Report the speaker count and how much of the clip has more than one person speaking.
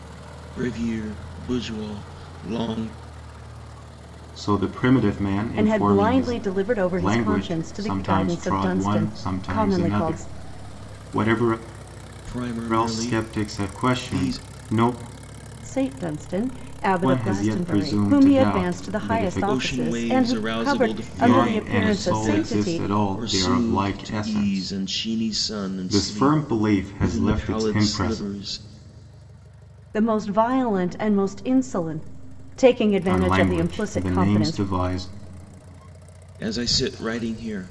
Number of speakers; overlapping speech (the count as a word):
three, about 46%